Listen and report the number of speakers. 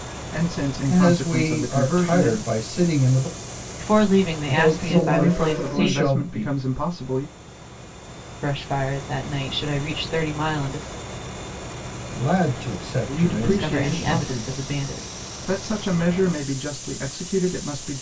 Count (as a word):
three